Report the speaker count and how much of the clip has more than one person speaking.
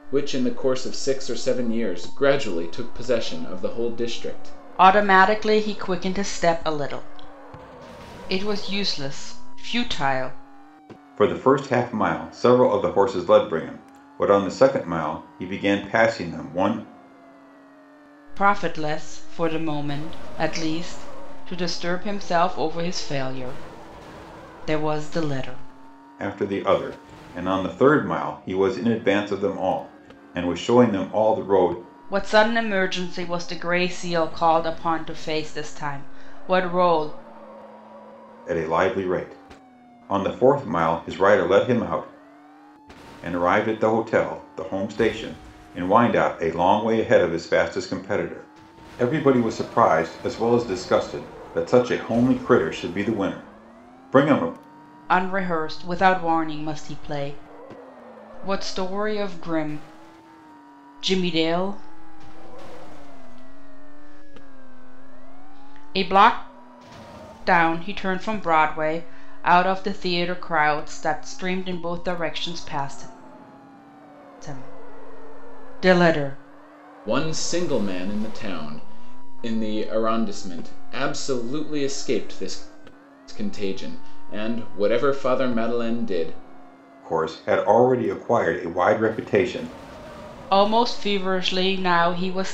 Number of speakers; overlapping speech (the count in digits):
3, no overlap